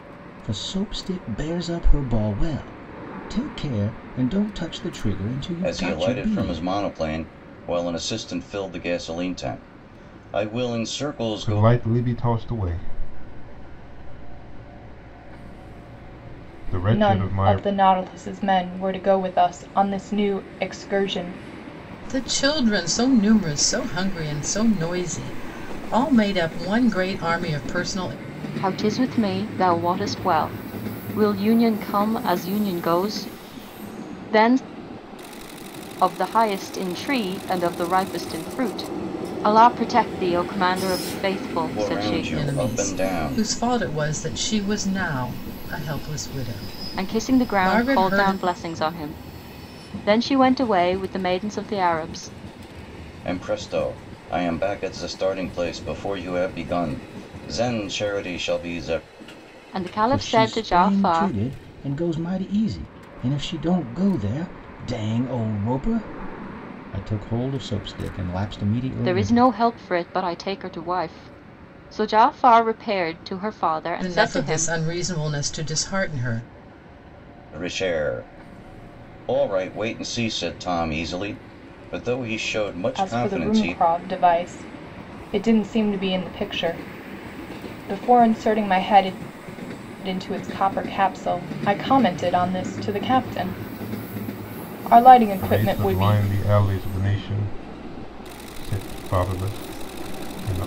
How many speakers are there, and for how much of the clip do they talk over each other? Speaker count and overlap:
6, about 9%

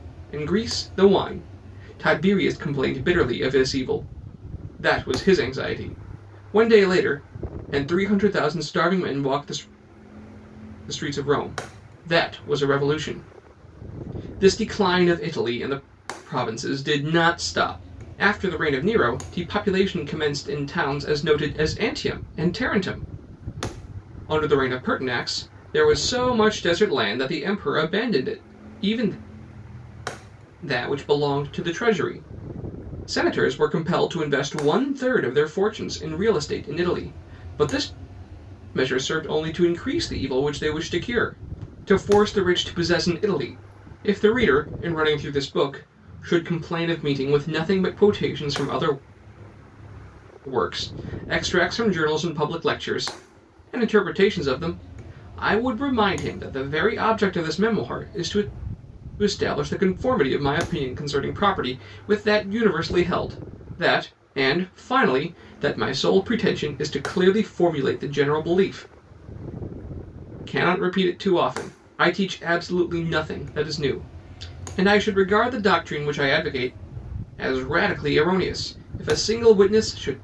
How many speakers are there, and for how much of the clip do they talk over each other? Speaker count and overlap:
1, no overlap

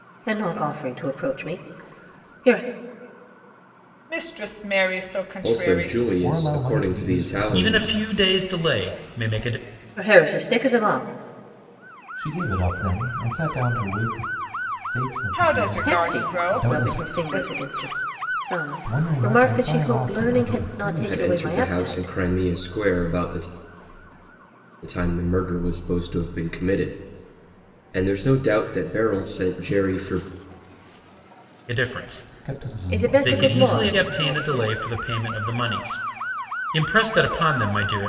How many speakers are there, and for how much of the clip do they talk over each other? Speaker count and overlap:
5, about 28%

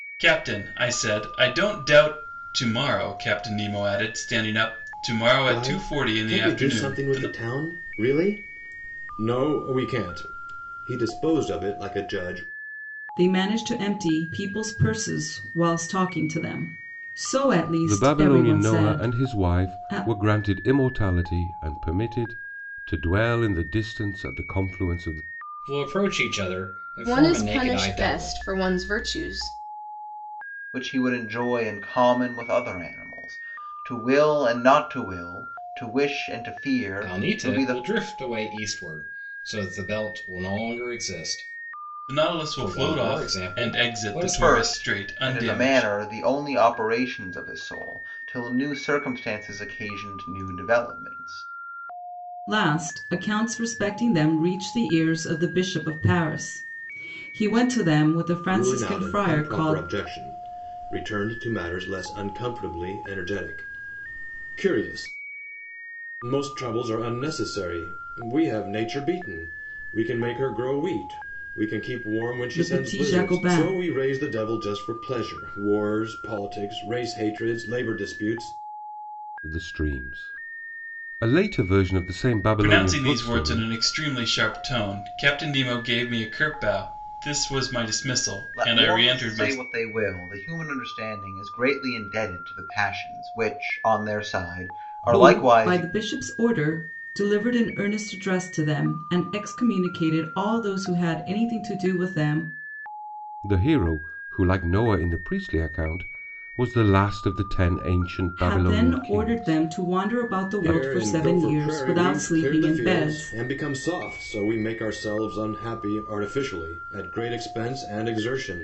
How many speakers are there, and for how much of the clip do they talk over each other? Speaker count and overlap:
7, about 18%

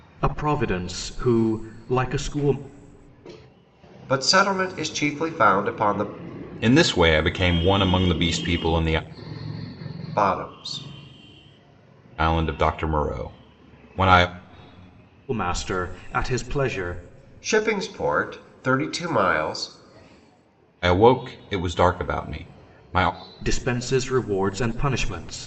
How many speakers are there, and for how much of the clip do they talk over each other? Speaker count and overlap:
3, no overlap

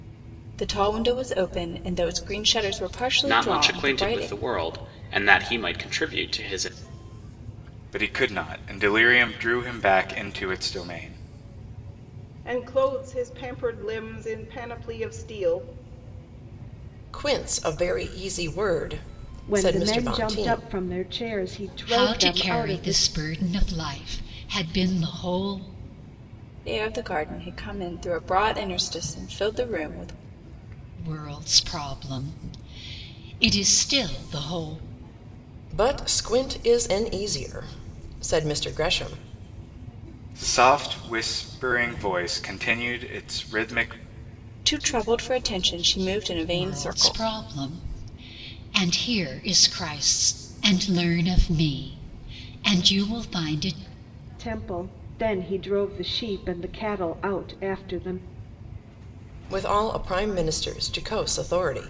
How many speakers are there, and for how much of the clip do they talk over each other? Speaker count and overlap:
7, about 7%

